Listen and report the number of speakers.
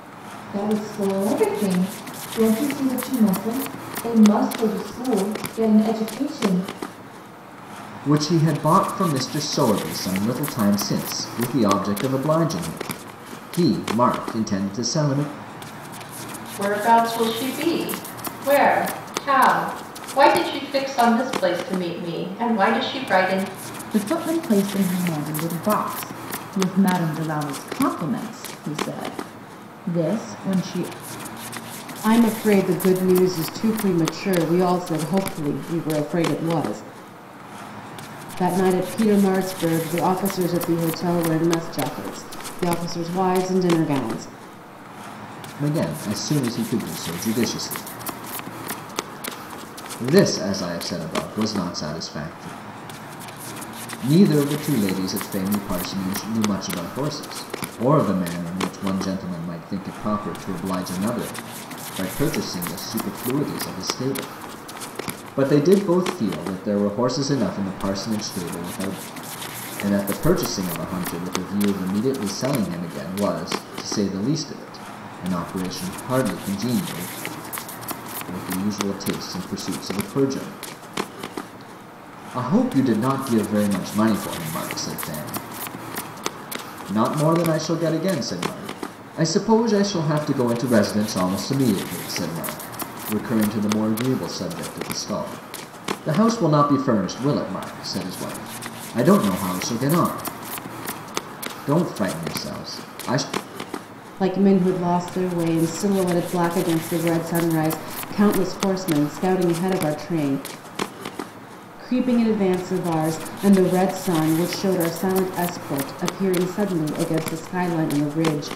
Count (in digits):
5